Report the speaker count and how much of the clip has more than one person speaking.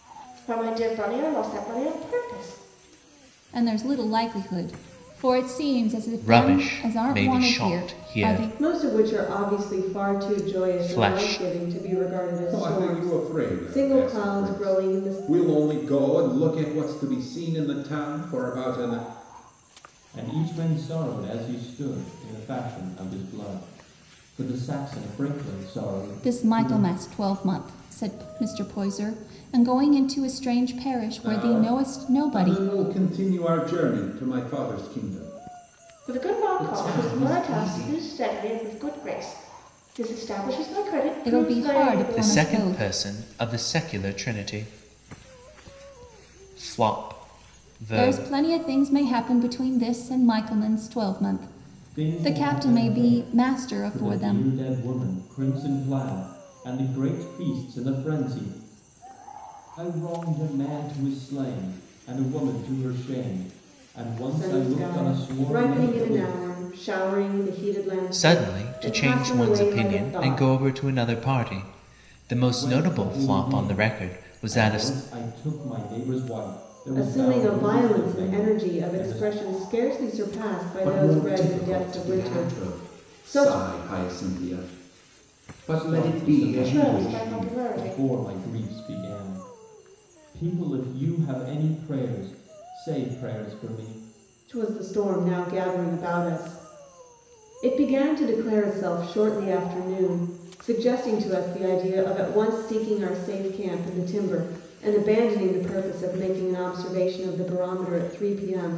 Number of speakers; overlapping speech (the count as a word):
six, about 29%